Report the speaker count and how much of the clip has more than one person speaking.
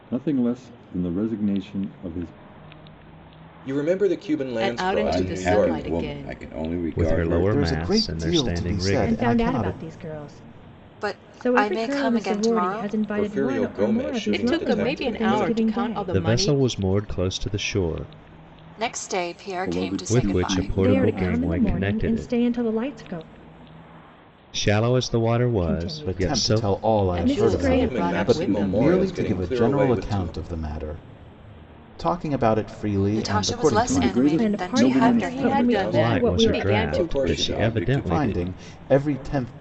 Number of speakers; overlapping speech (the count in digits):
8, about 58%